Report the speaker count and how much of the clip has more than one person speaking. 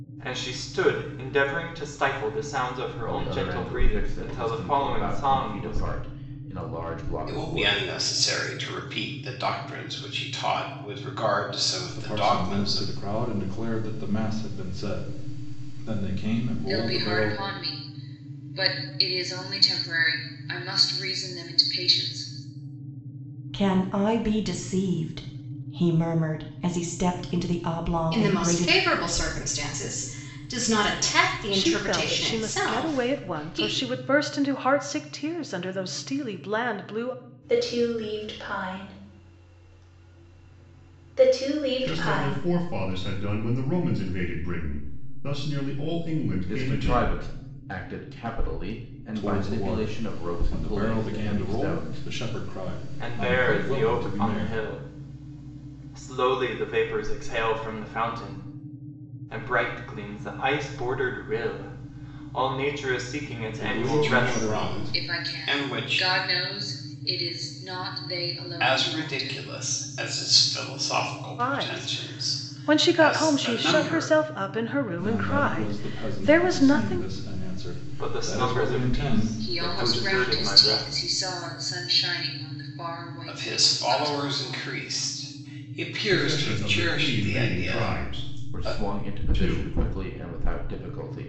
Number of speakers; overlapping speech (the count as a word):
ten, about 34%